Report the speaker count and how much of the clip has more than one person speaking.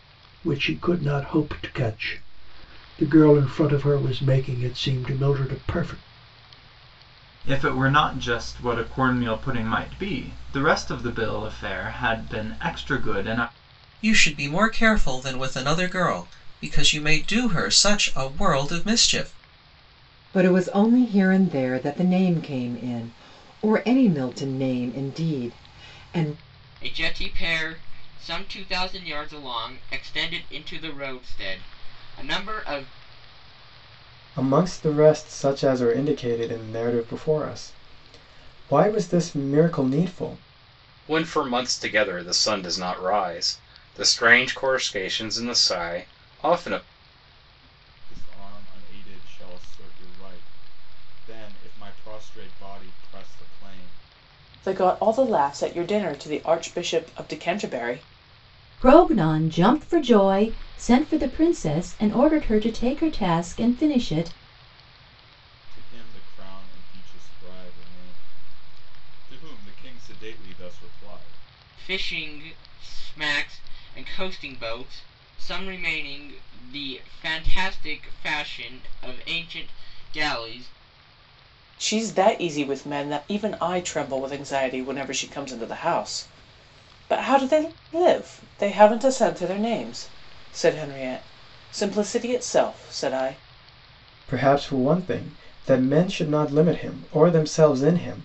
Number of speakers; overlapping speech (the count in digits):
10, no overlap